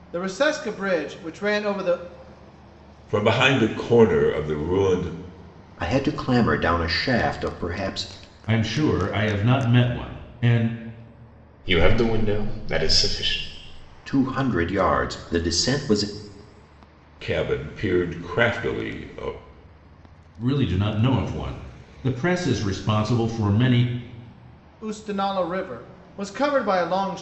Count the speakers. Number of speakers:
5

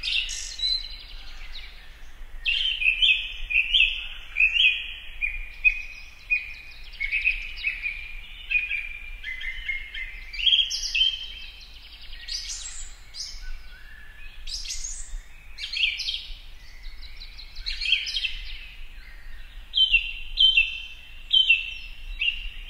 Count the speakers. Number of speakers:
0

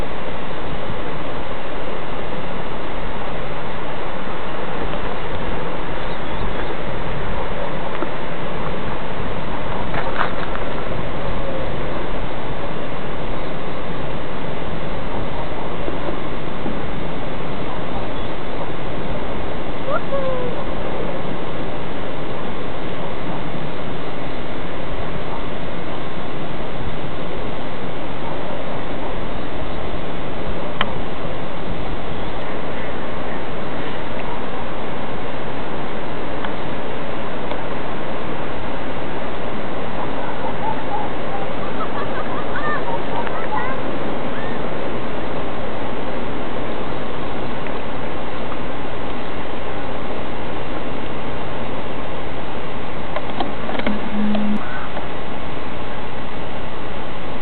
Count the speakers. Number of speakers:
0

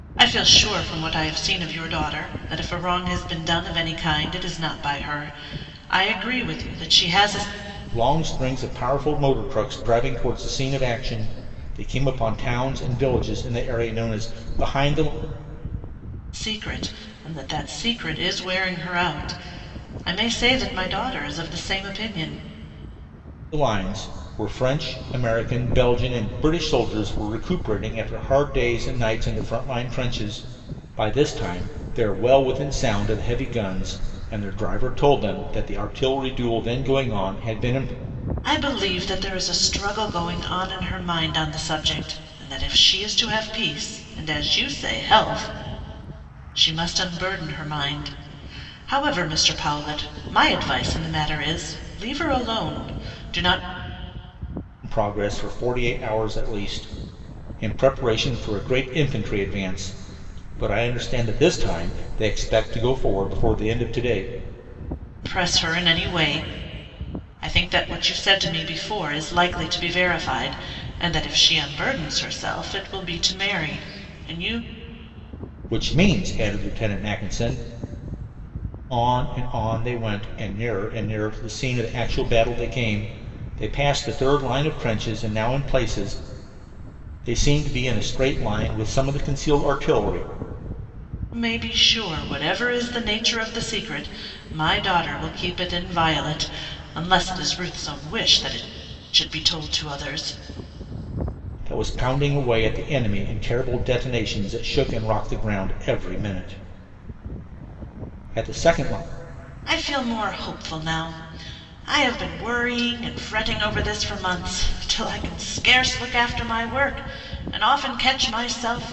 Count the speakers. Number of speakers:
2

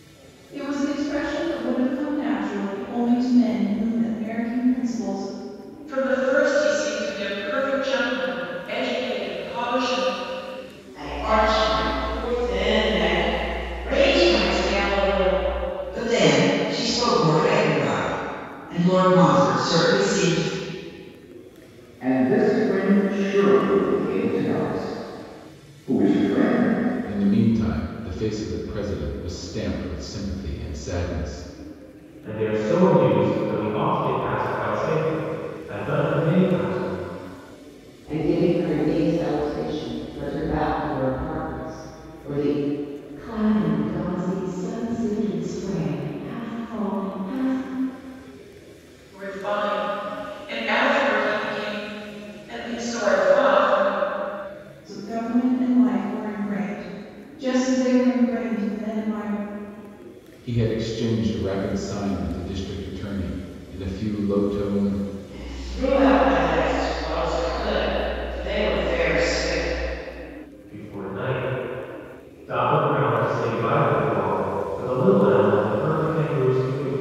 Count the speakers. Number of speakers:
9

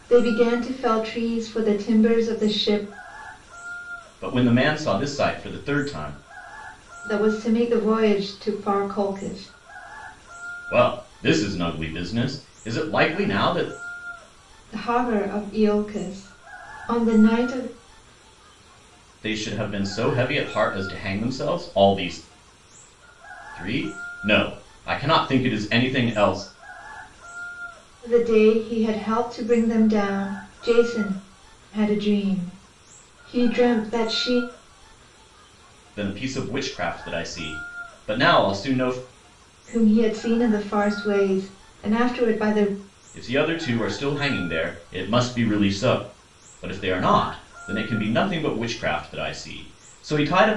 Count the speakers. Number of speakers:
2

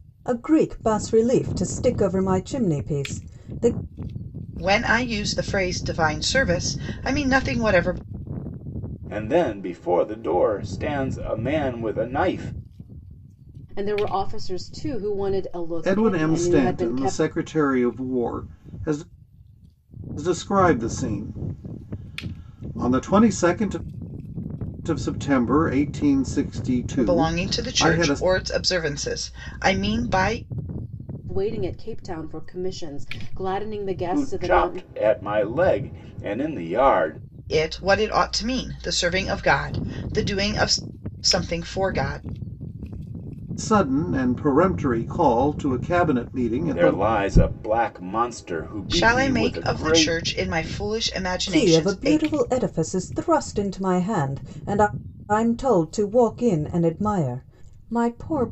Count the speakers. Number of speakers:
5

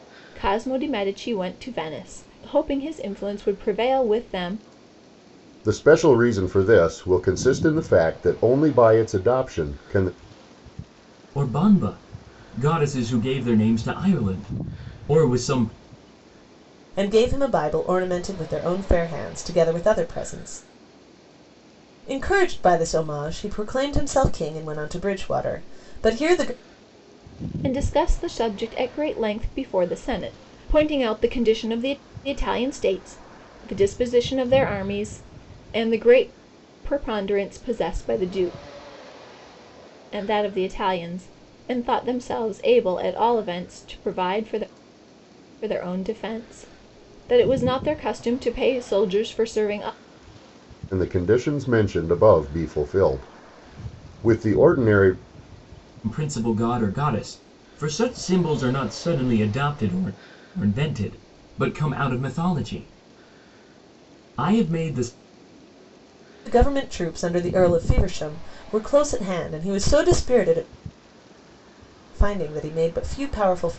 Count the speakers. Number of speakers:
4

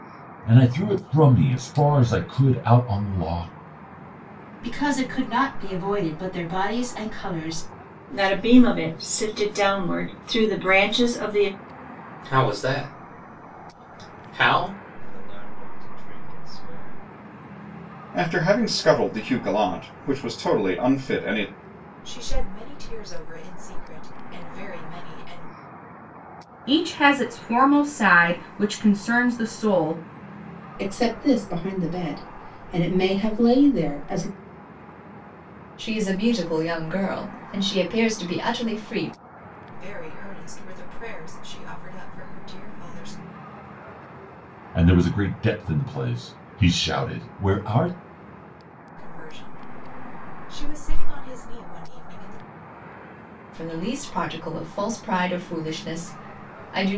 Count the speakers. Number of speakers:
10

